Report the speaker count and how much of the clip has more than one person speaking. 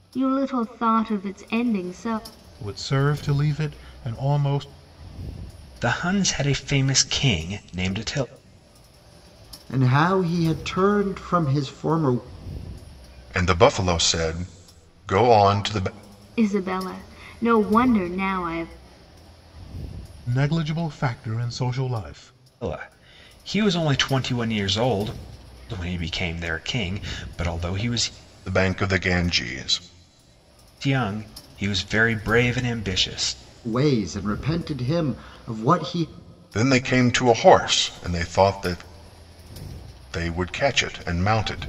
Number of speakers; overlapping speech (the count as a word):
five, no overlap